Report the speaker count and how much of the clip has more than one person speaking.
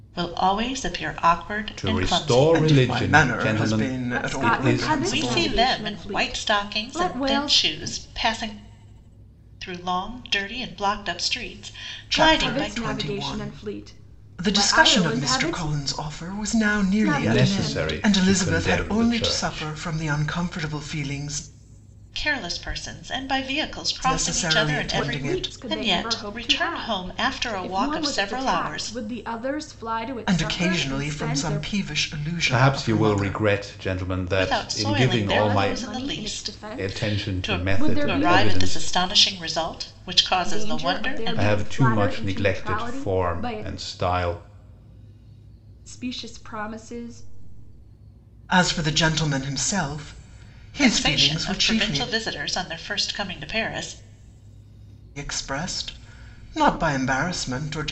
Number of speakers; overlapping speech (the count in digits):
4, about 48%